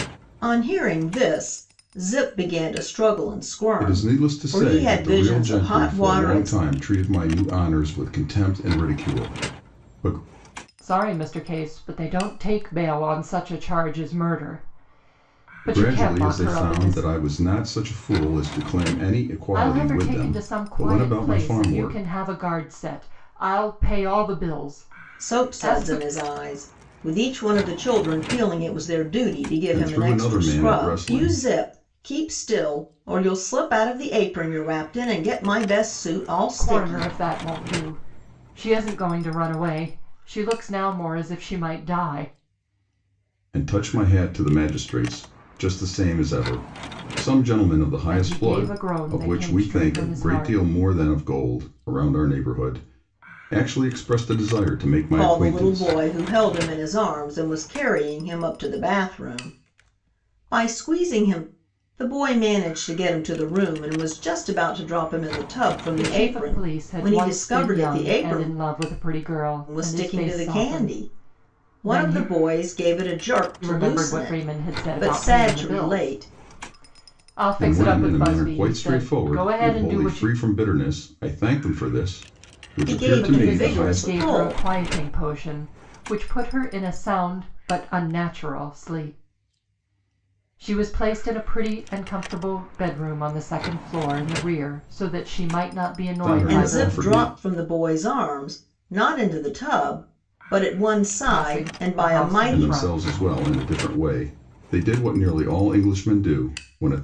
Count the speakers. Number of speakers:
3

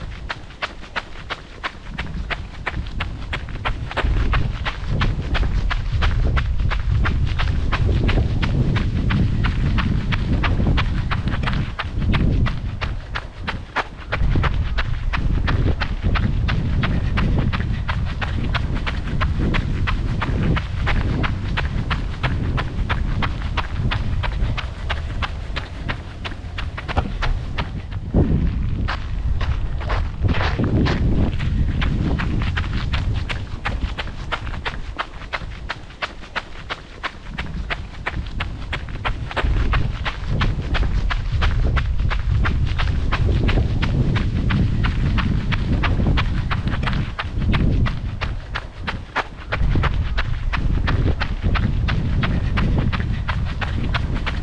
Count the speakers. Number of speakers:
0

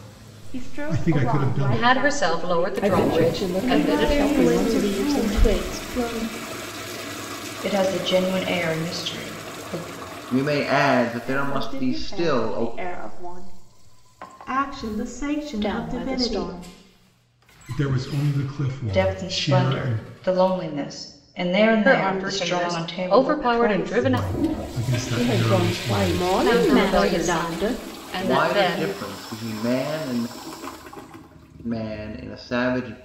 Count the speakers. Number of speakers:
8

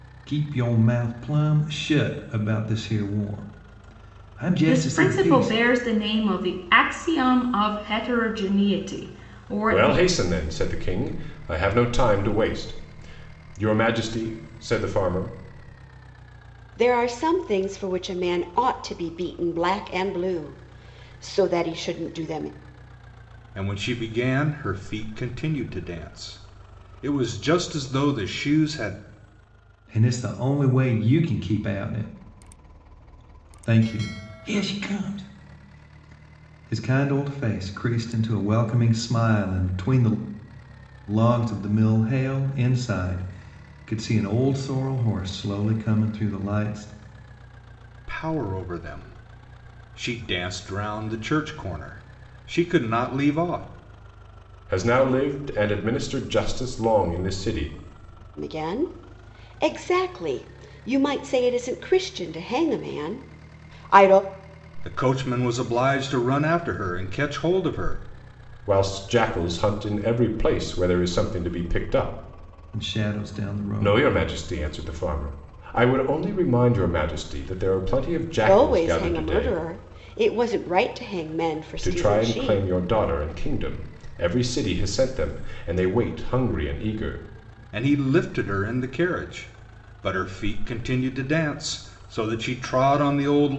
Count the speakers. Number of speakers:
5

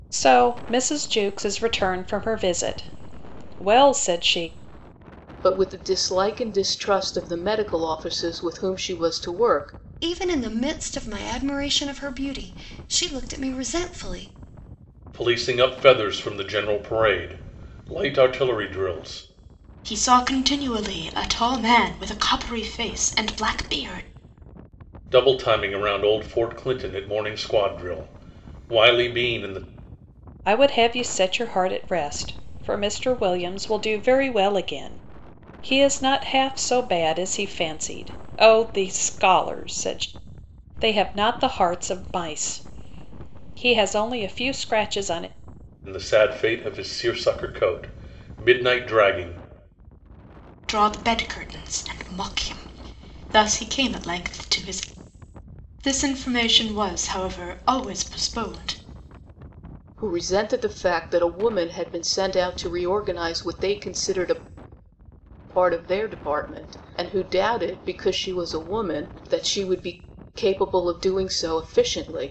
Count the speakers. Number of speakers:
5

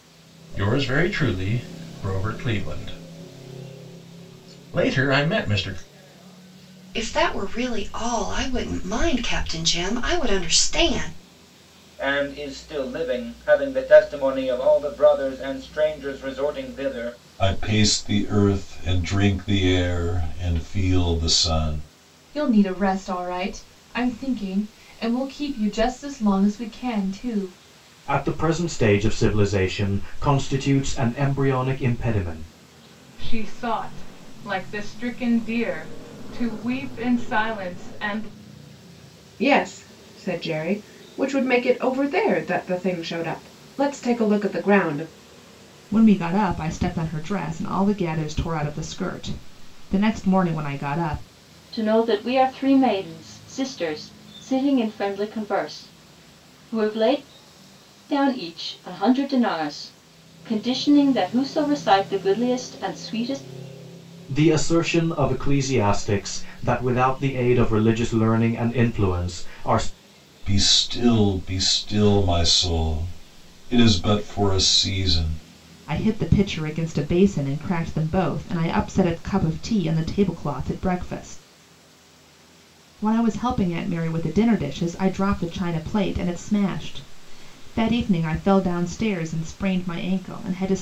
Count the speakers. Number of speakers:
10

